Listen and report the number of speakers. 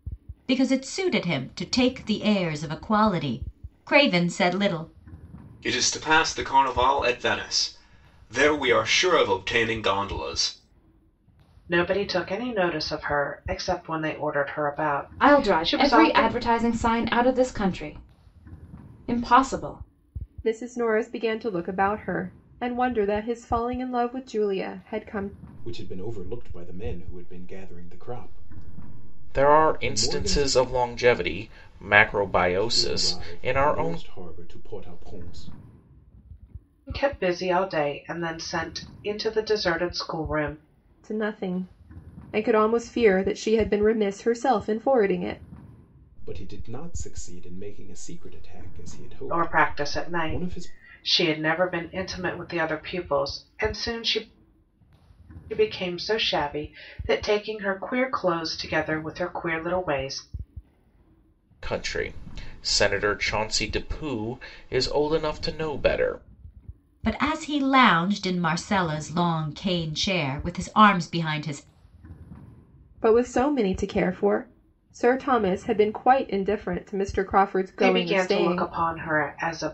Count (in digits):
7